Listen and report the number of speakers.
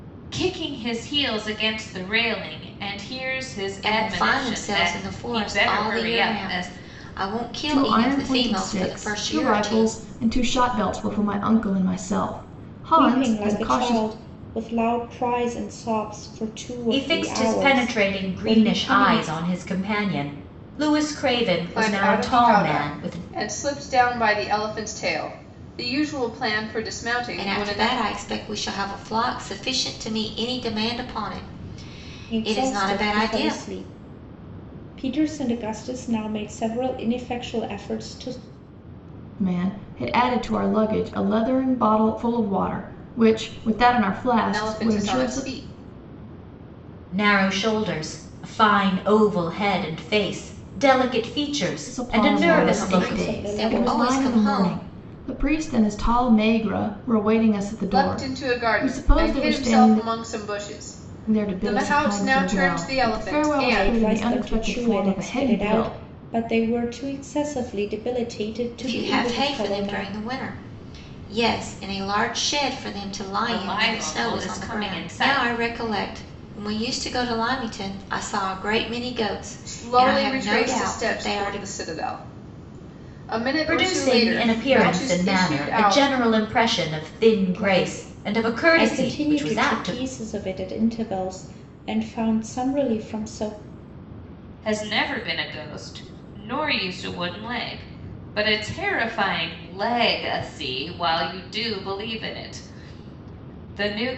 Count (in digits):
6